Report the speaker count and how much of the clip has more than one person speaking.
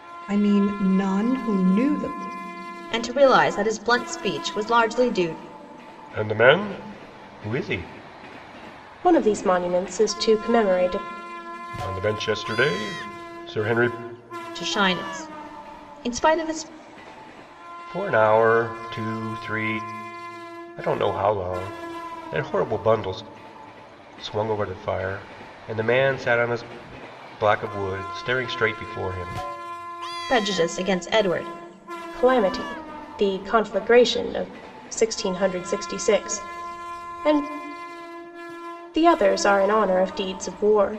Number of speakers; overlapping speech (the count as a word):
four, no overlap